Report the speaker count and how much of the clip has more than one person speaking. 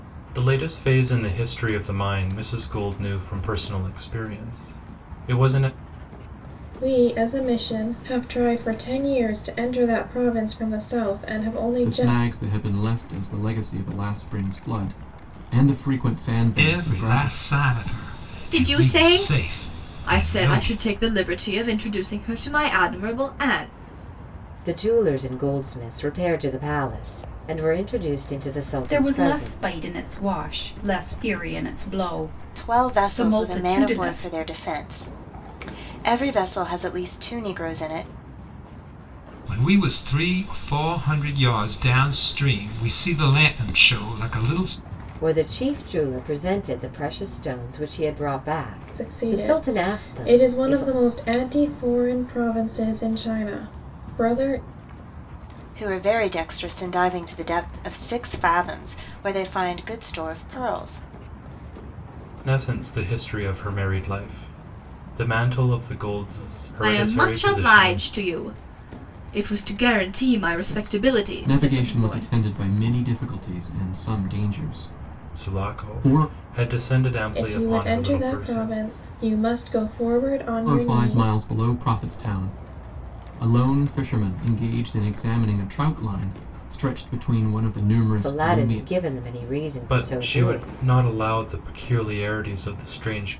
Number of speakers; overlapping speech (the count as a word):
eight, about 18%